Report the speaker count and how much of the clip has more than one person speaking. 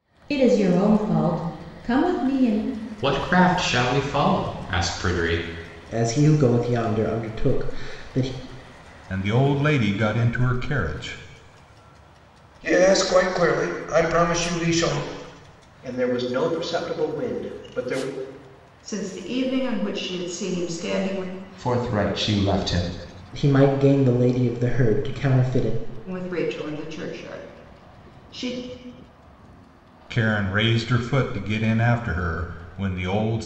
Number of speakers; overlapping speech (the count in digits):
8, no overlap